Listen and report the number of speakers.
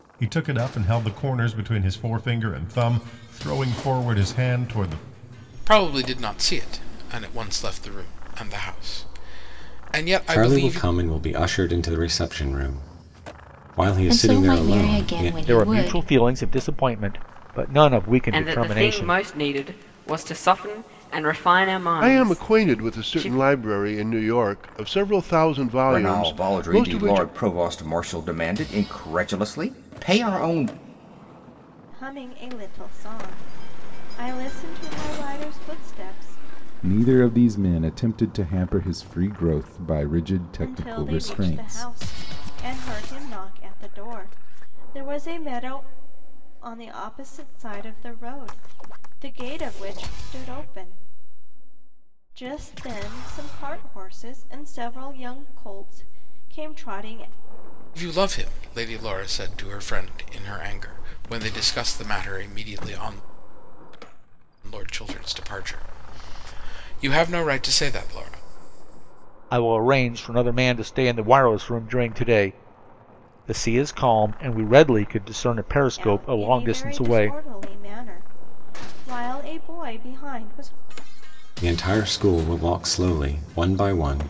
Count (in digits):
10